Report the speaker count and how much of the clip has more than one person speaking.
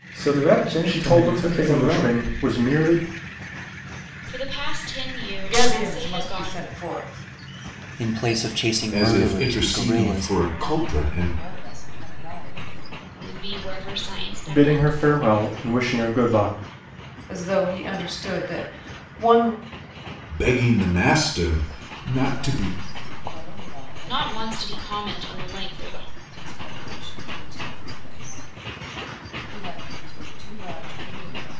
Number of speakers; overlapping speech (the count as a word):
seven, about 20%